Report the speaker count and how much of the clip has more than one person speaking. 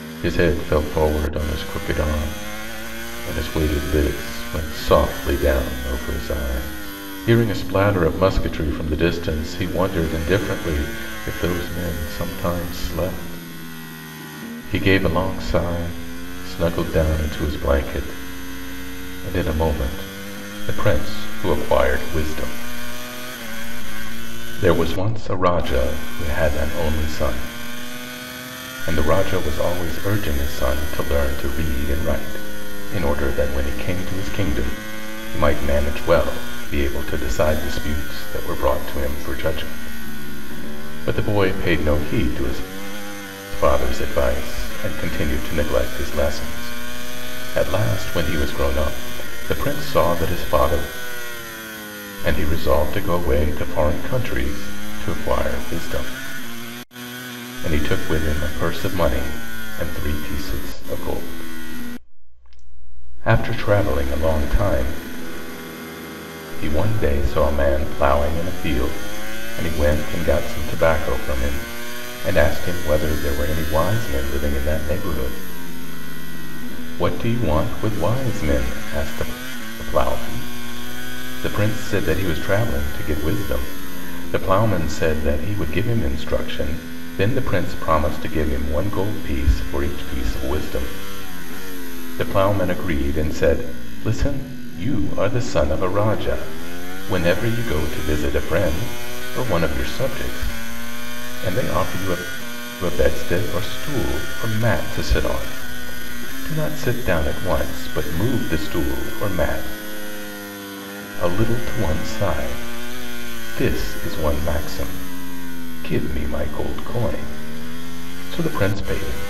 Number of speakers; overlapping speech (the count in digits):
1, no overlap